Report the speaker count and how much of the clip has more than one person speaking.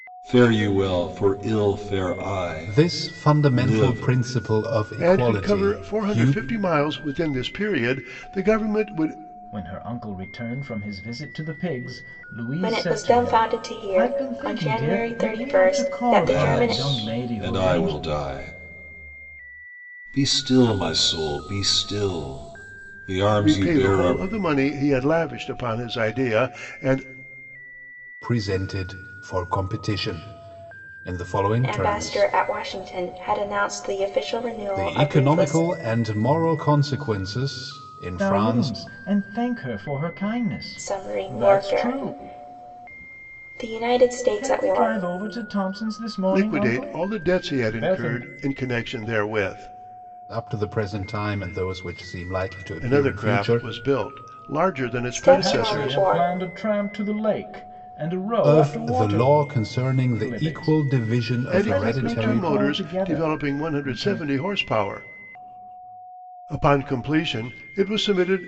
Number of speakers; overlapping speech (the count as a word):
five, about 32%